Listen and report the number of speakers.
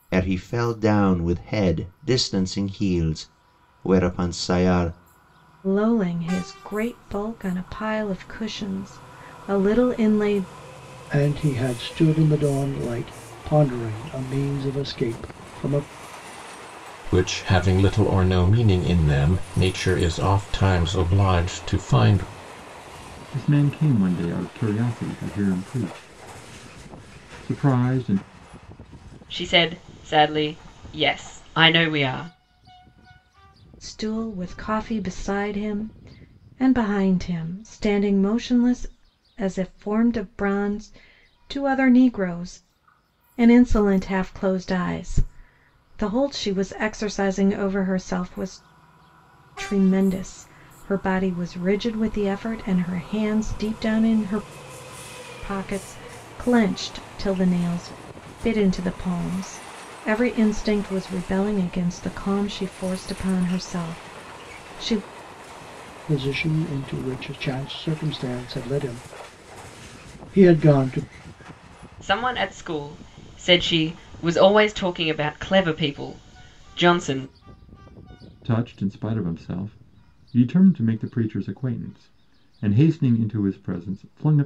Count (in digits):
6